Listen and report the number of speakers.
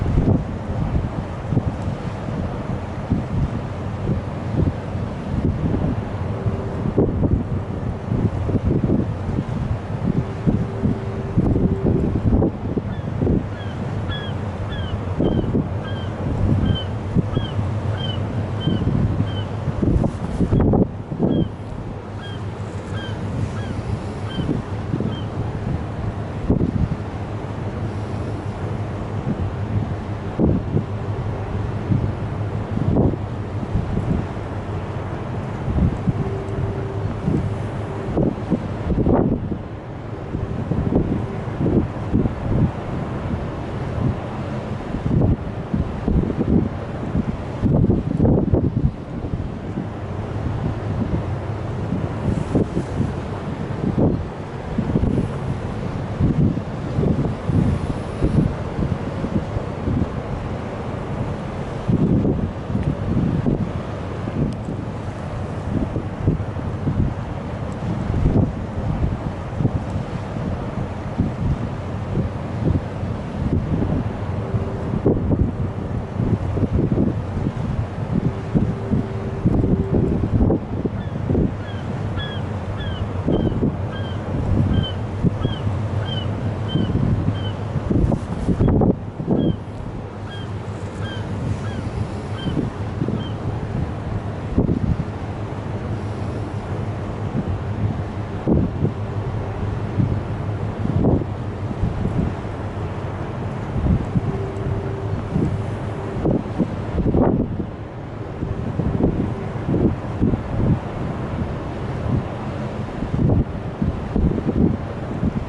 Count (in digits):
0